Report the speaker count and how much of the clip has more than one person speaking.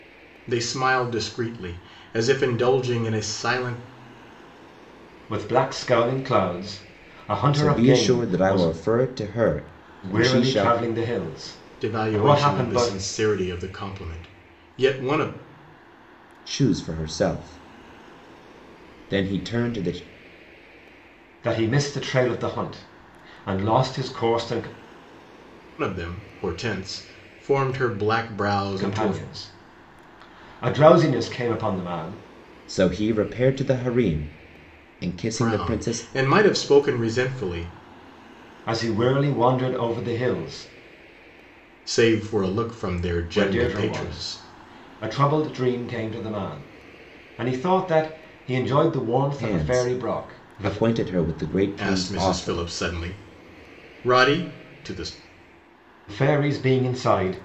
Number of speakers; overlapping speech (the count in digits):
3, about 14%